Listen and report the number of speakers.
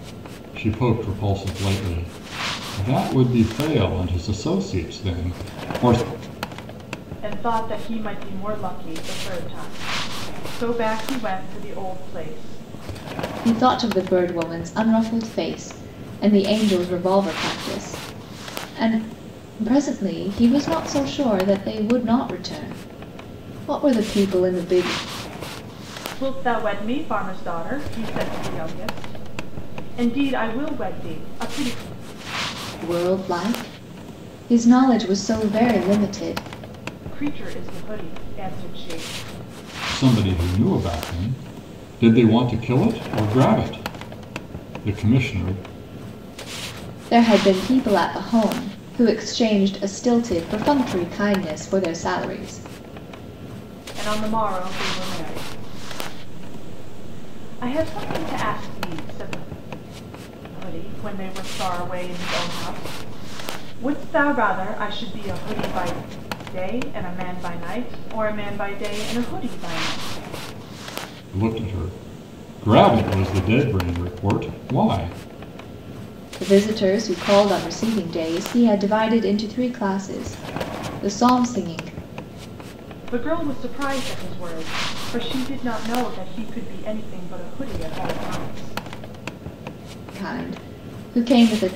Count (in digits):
3